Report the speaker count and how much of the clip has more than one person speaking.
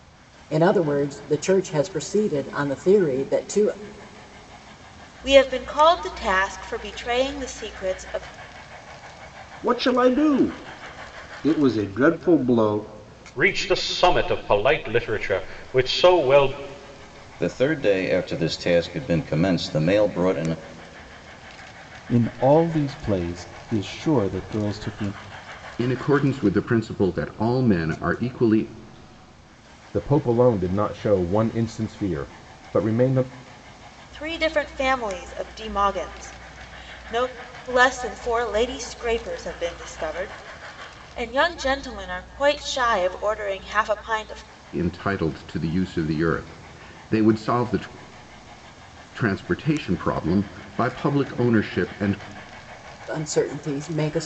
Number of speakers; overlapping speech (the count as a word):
eight, no overlap